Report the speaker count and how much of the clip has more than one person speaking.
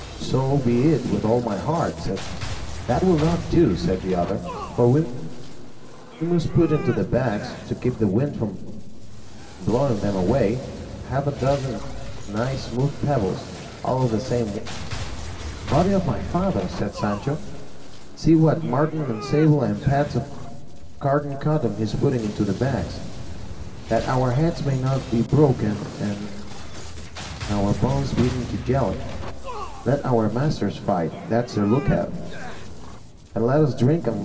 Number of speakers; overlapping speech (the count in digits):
1, no overlap